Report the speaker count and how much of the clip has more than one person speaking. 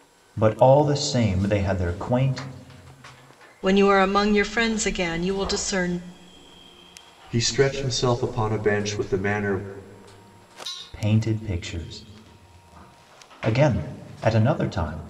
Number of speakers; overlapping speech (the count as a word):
three, no overlap